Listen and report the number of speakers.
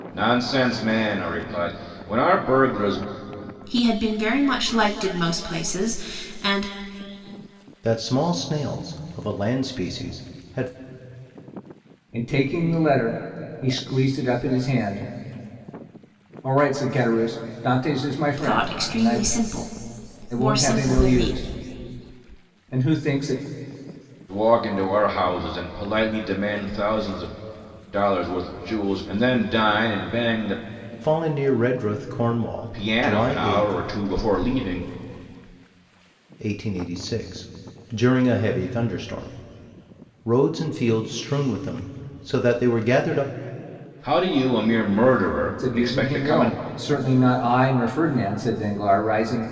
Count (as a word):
four